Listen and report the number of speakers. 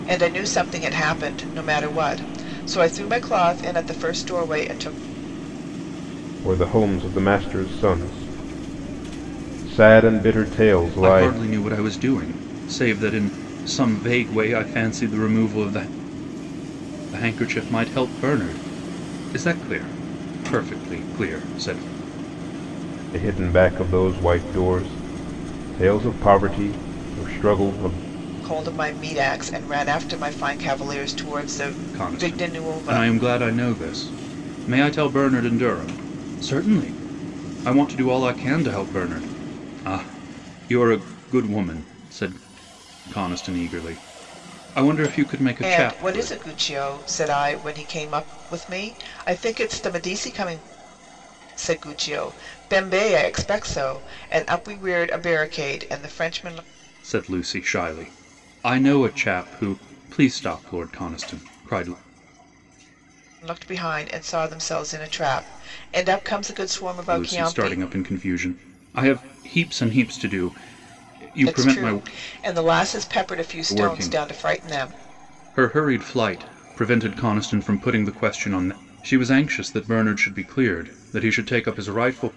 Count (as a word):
three